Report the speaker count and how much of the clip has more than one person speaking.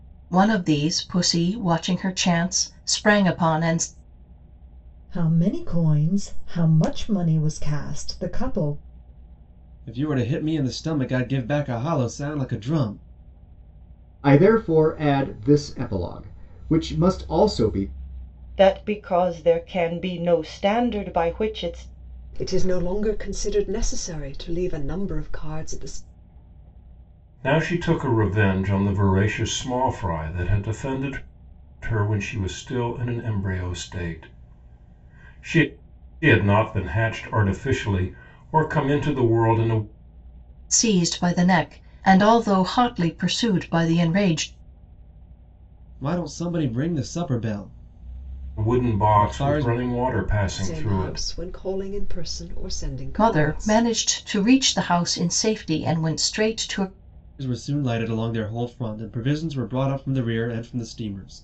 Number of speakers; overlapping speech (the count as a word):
seven, about 4%